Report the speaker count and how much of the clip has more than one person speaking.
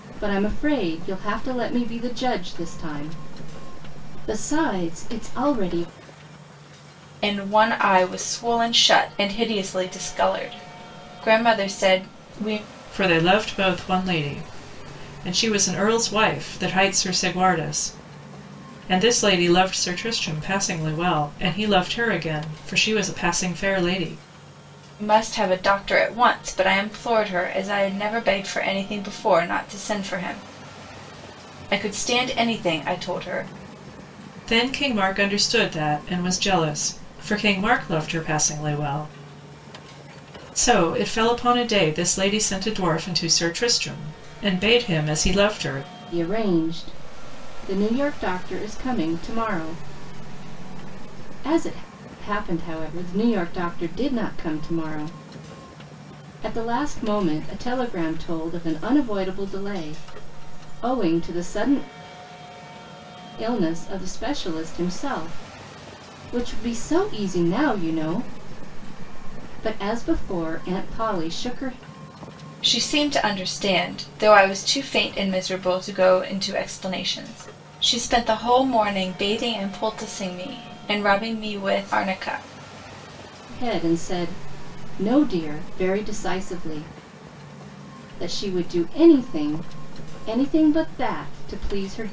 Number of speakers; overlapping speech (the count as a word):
three, no overlap